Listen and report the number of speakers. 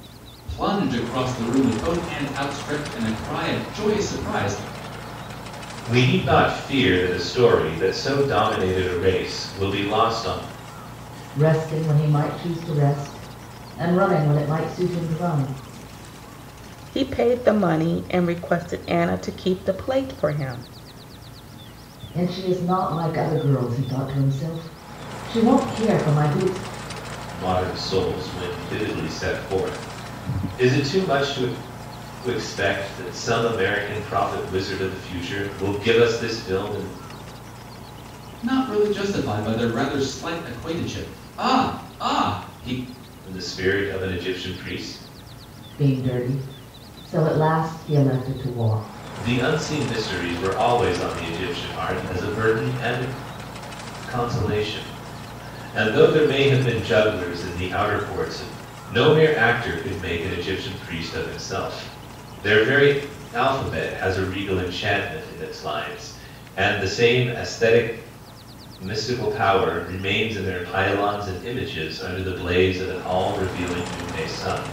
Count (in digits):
4